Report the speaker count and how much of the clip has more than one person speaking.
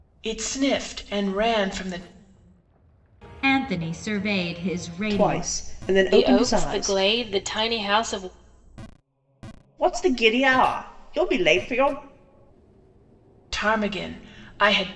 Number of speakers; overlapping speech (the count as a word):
four, about 10%